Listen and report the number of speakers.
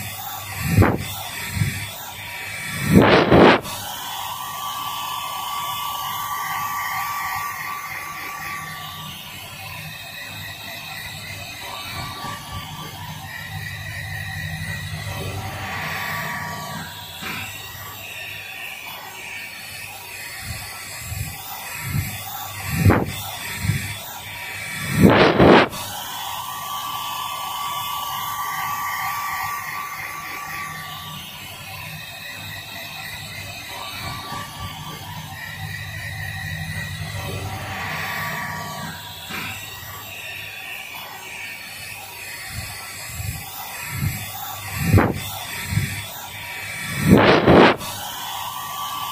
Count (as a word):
zero